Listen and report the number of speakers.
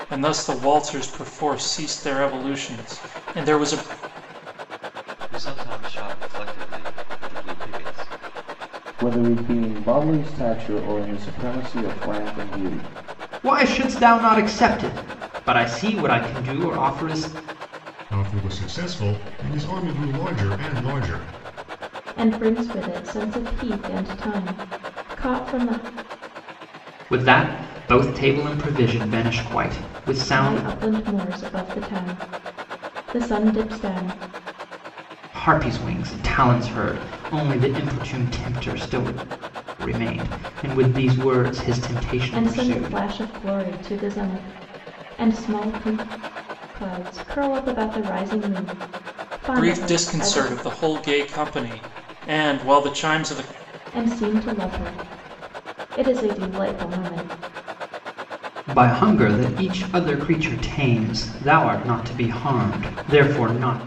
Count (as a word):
six